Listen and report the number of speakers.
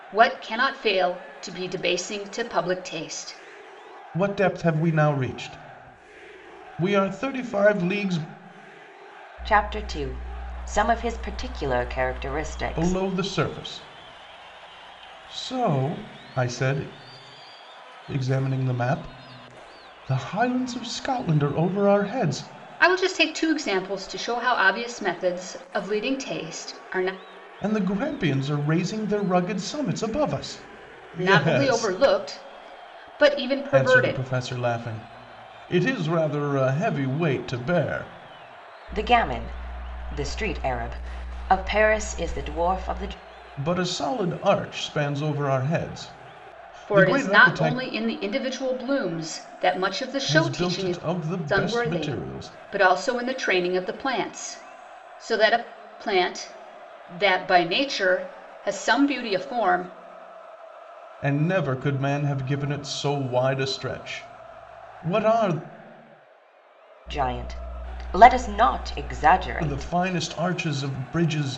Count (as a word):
three